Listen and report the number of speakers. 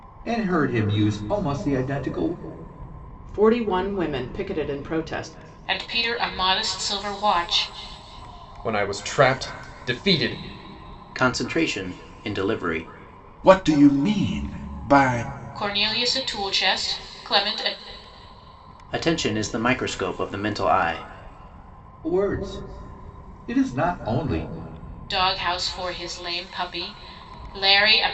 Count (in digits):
6